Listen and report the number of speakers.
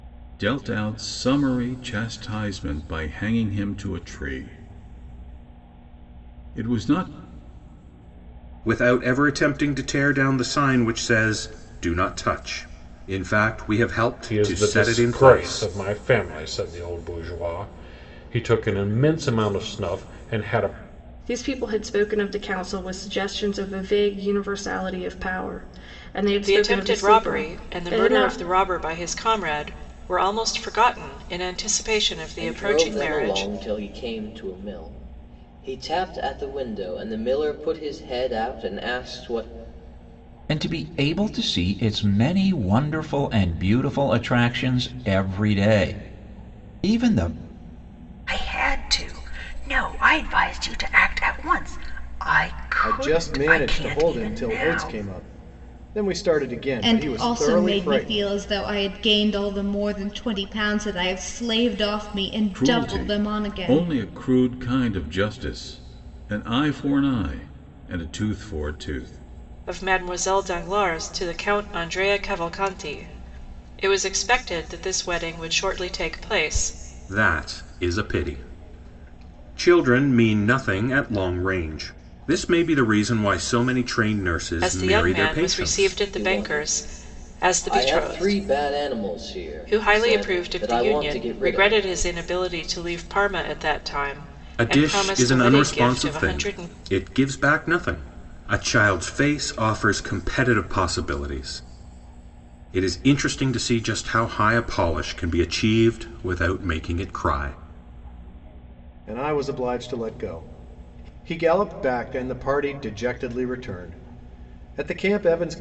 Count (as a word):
ten